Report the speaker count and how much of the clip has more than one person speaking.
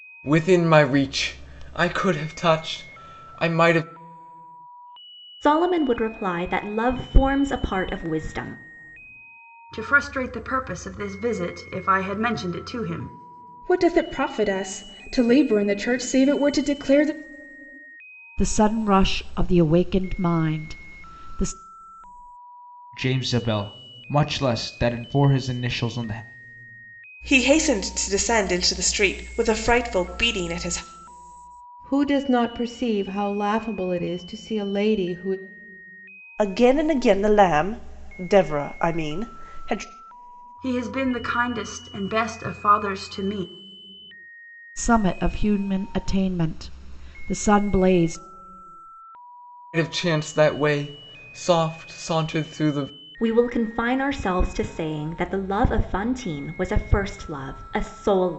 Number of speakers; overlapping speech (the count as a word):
nine, no overlap